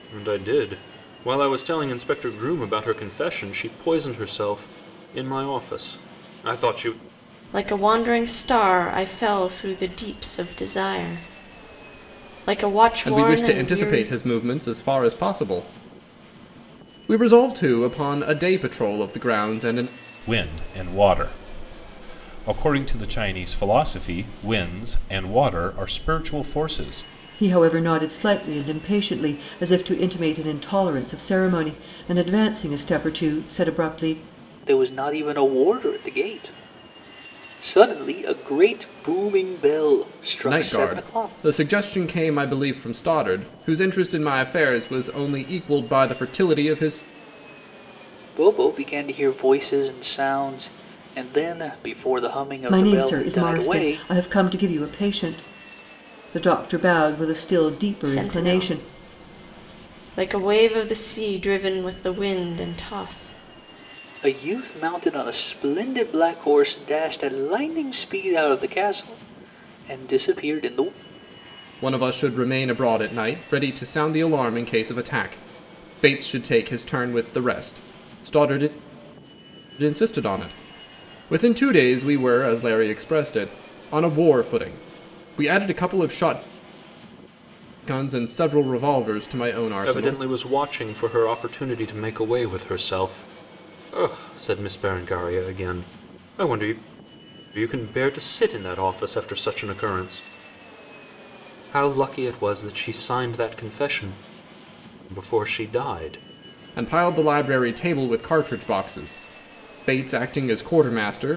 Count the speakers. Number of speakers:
6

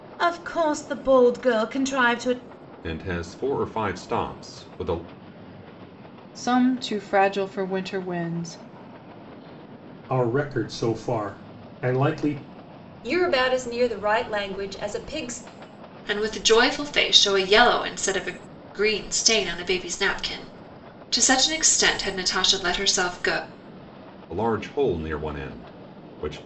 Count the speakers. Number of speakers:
6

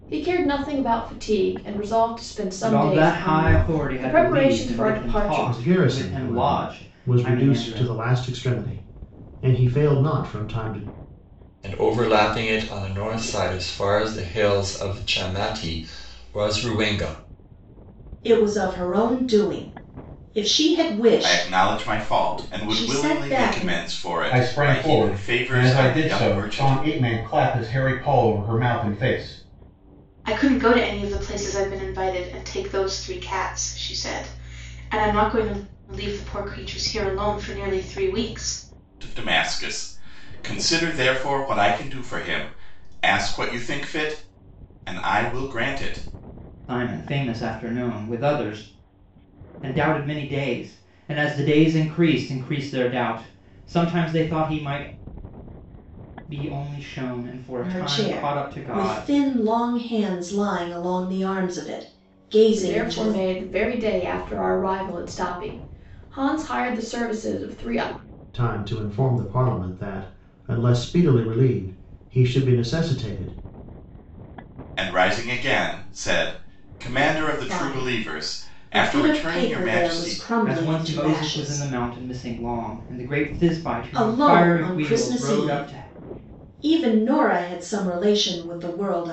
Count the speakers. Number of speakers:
8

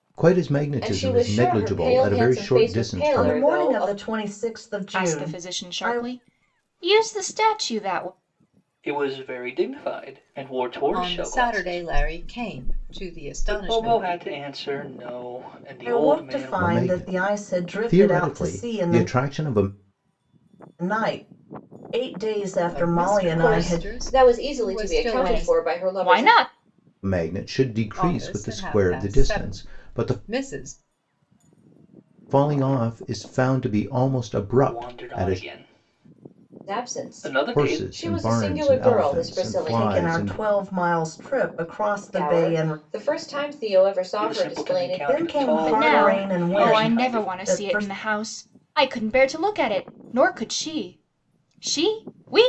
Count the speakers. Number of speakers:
6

